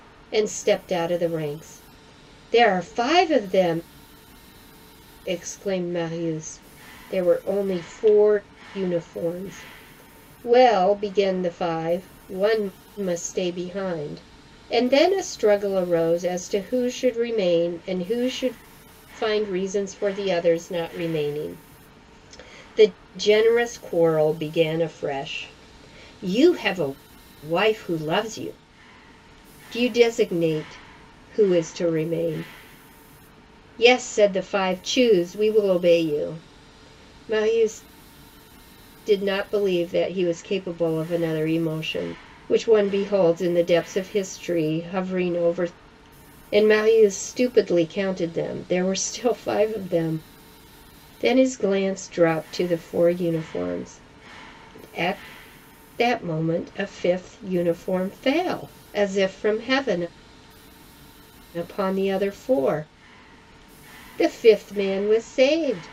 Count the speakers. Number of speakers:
1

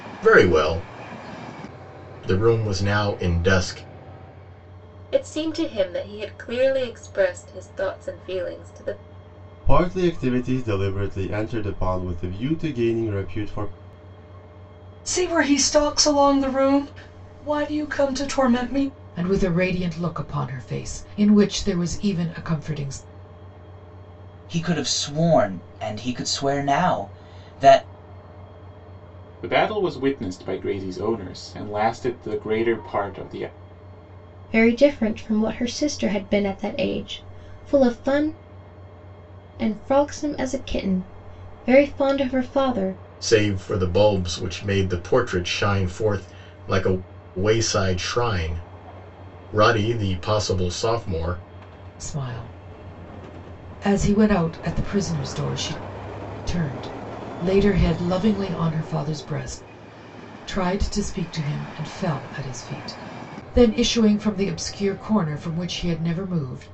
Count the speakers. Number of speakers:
8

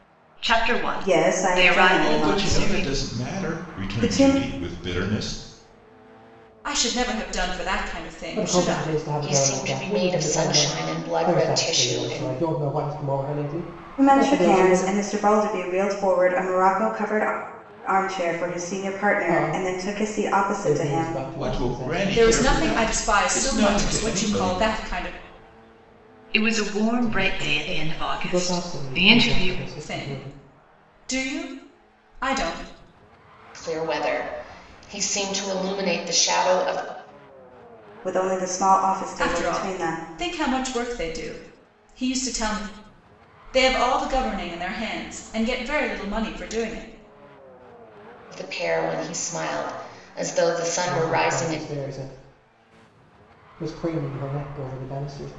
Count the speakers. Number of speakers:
6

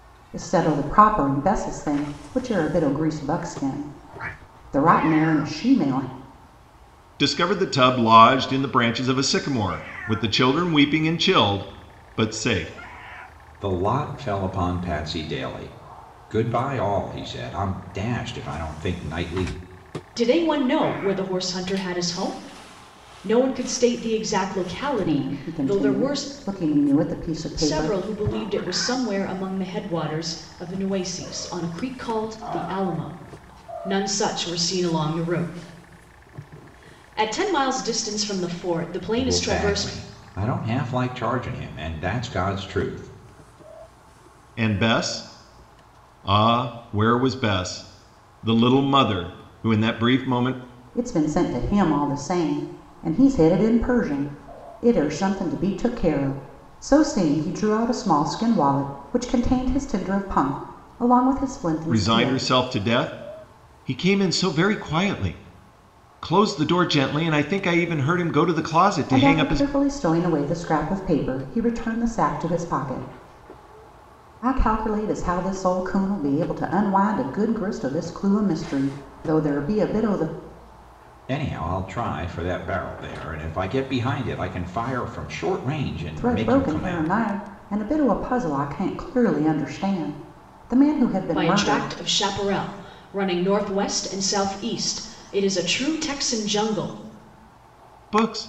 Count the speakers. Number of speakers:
4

